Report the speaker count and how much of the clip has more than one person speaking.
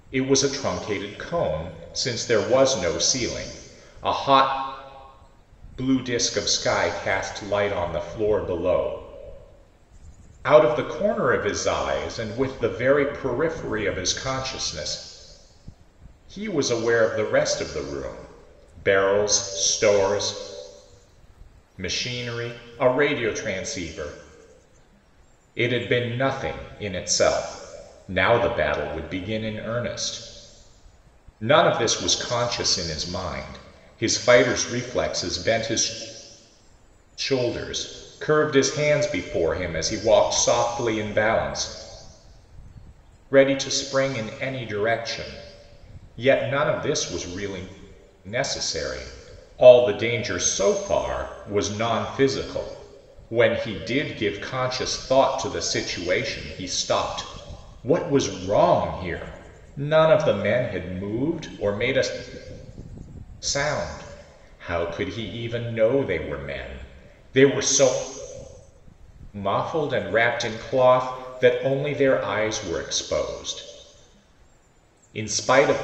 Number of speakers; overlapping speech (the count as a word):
one, no overlap